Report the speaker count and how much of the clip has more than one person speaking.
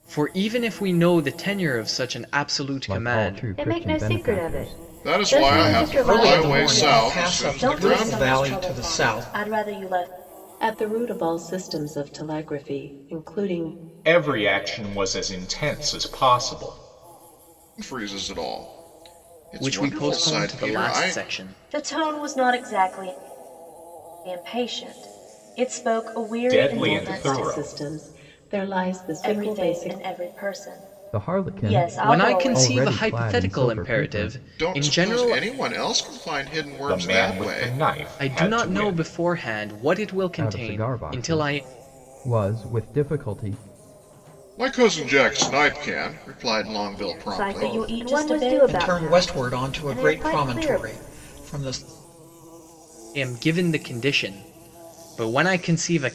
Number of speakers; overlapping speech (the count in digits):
8, about 39%